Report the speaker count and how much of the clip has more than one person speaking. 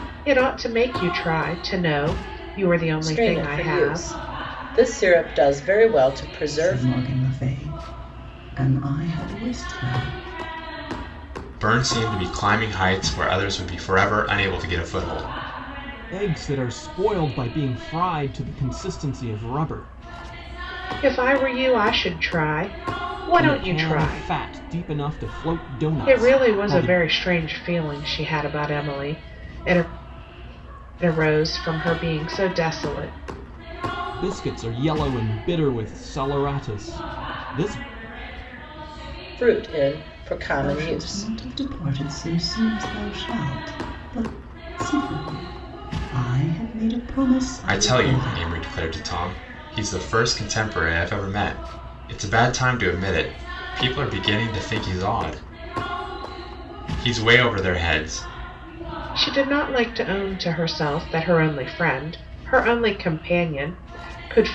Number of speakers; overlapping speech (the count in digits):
5, about 8%